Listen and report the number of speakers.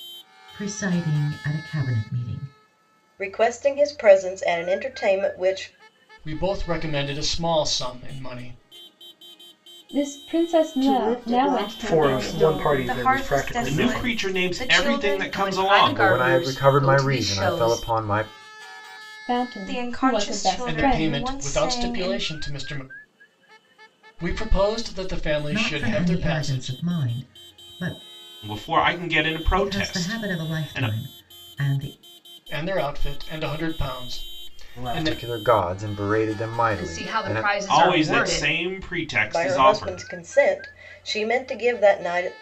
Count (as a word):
ten